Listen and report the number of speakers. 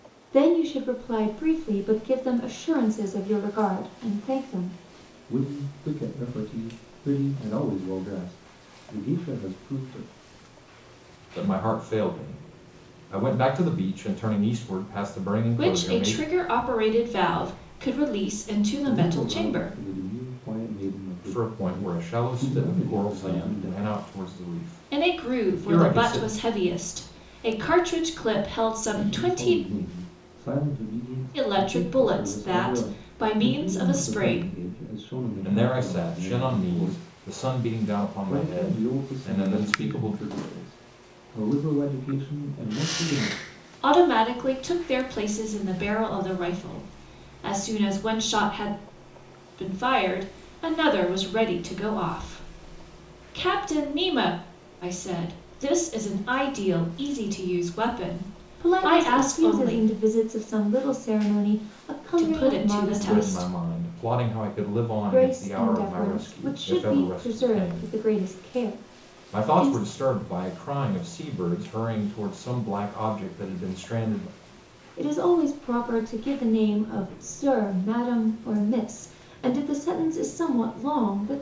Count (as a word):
four